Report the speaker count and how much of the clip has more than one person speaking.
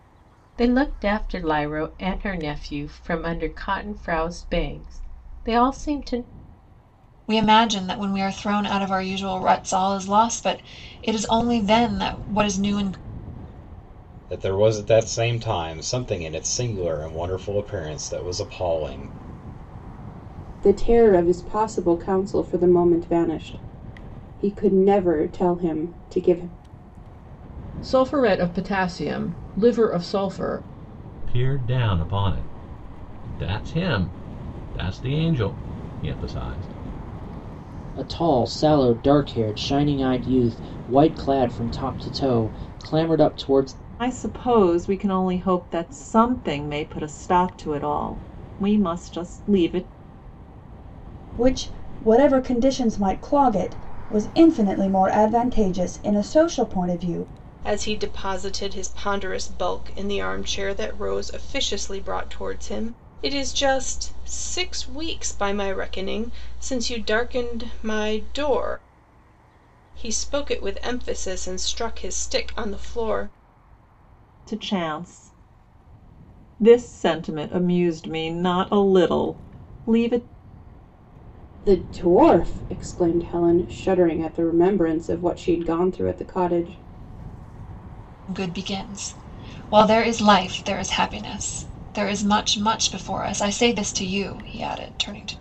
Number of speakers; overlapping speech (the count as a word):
ten, no overlap